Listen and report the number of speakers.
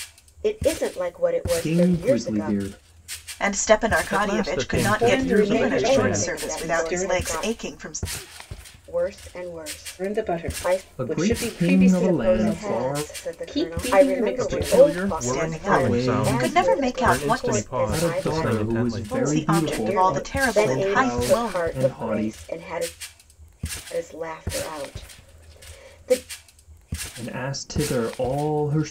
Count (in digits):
5